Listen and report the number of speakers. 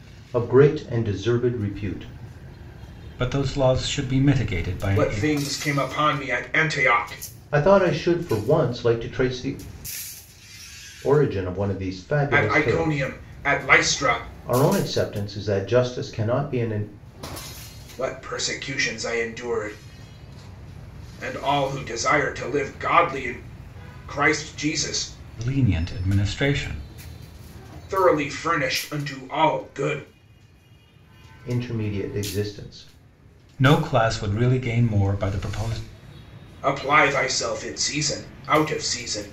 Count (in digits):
3